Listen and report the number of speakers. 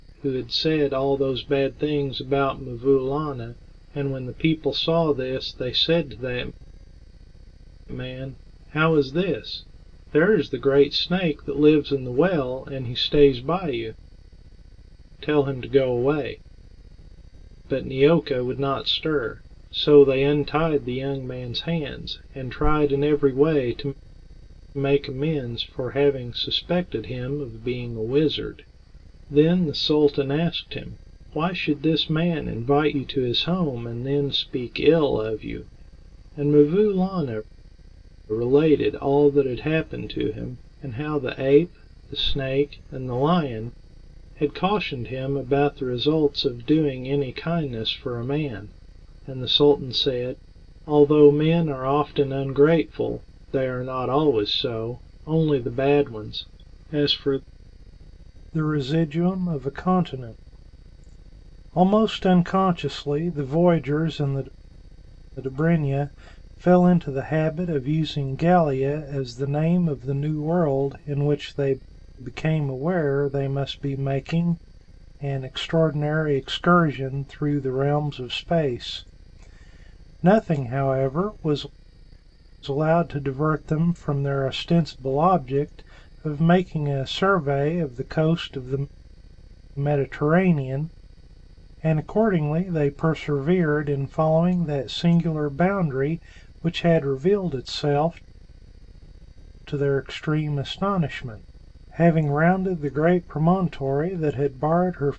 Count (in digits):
1